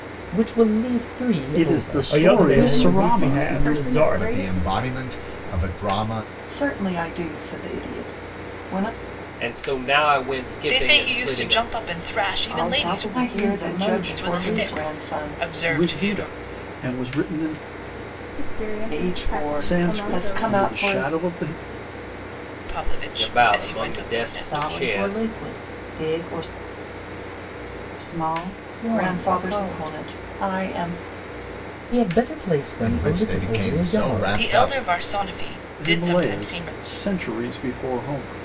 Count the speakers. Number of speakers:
nine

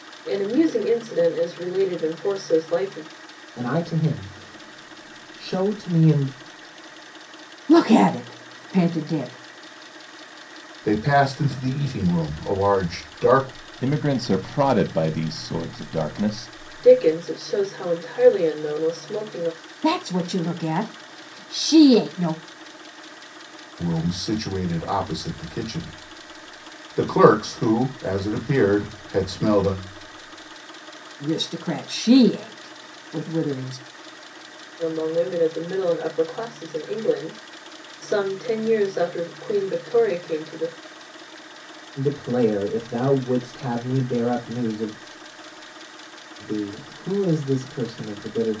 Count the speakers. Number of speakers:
five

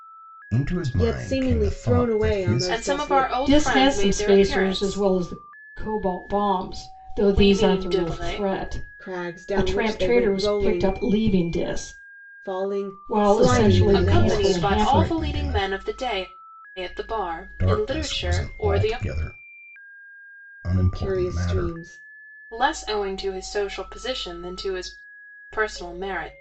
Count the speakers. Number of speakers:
four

